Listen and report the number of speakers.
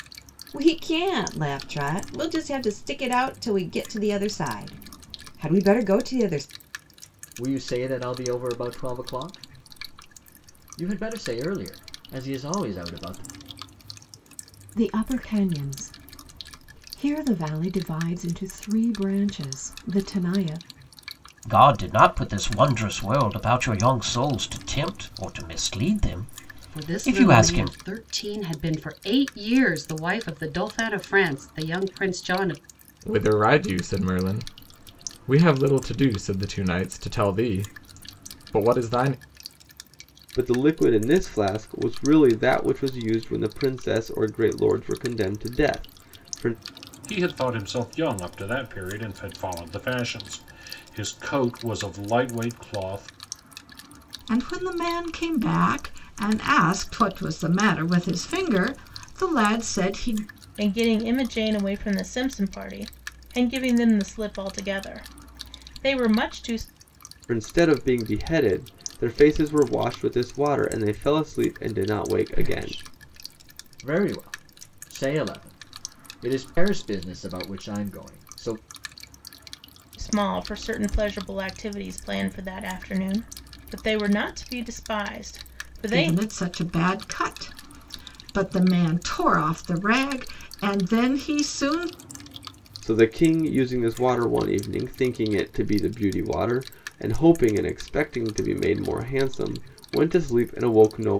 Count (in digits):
10